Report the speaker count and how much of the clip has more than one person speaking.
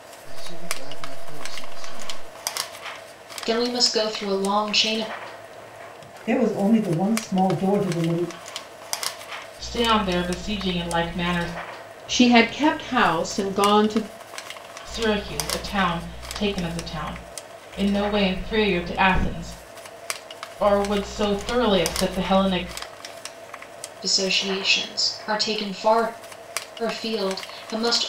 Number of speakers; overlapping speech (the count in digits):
5, no overlap